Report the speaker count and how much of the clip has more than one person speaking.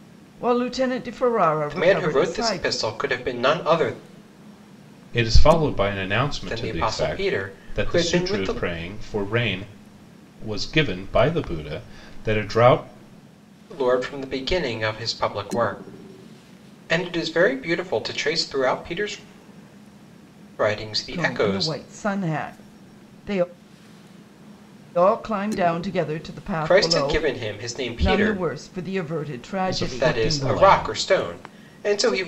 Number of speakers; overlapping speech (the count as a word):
three, about 19%